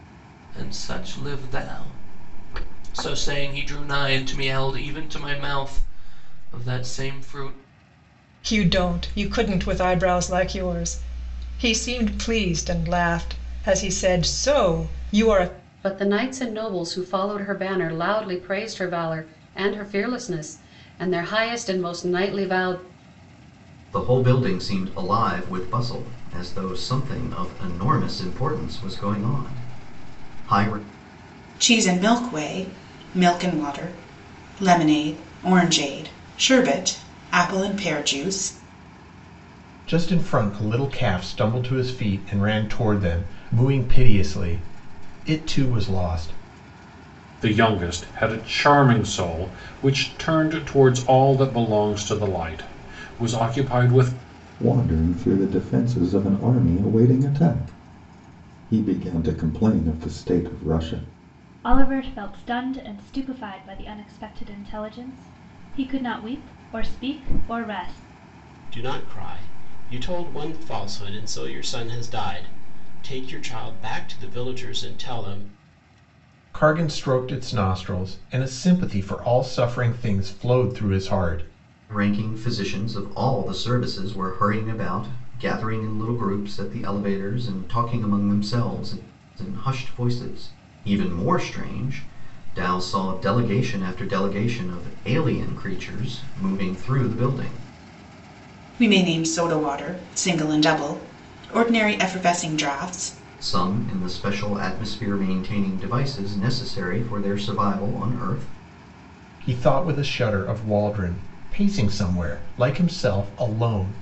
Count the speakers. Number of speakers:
ten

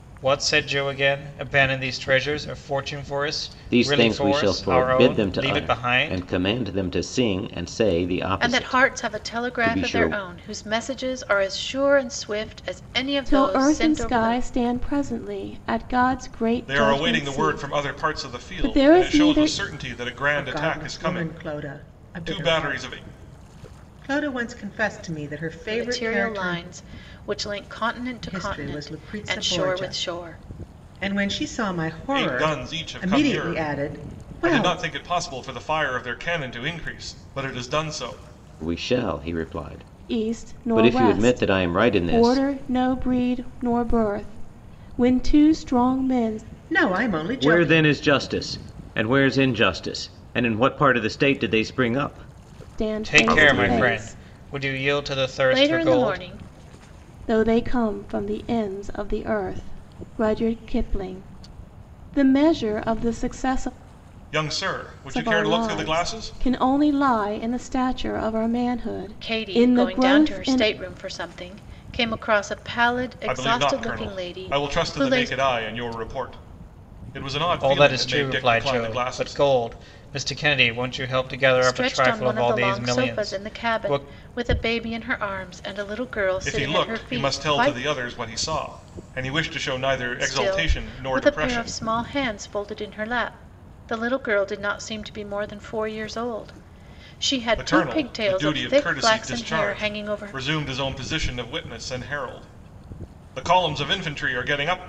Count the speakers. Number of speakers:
six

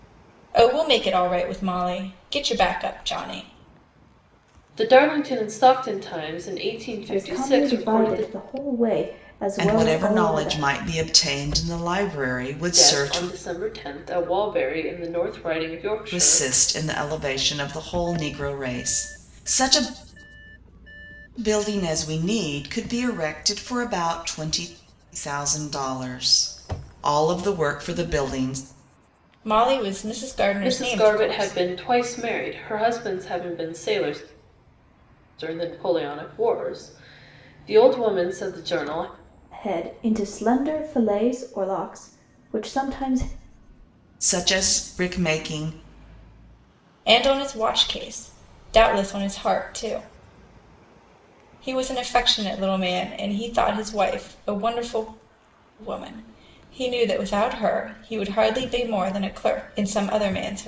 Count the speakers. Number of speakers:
four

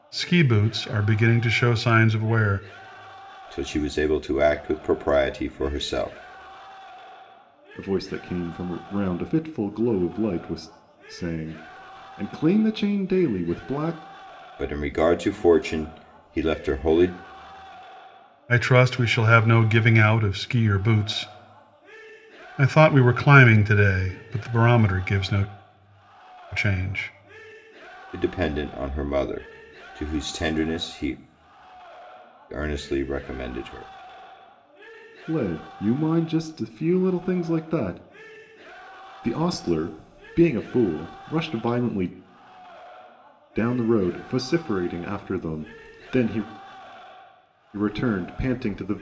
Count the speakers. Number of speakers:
three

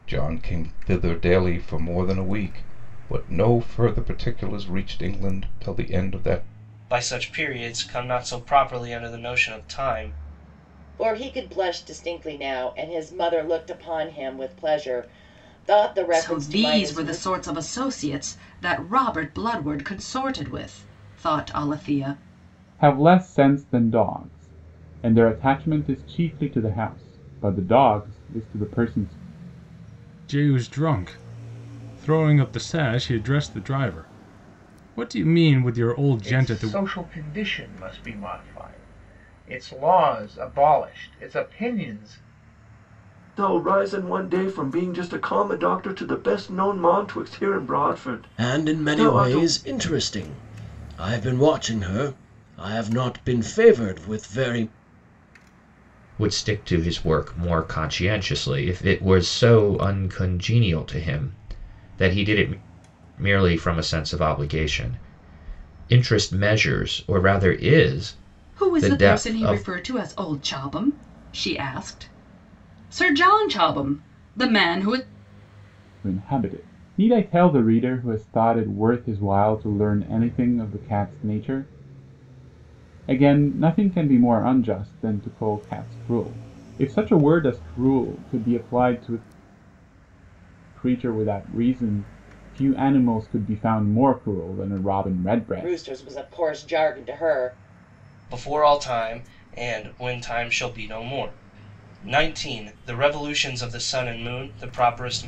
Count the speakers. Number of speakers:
ten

